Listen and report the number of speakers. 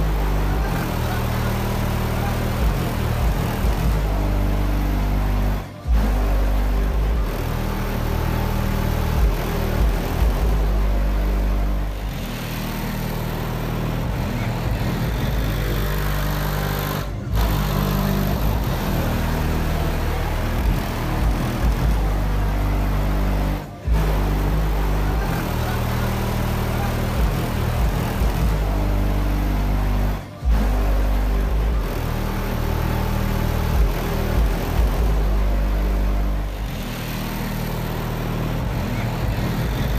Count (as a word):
zero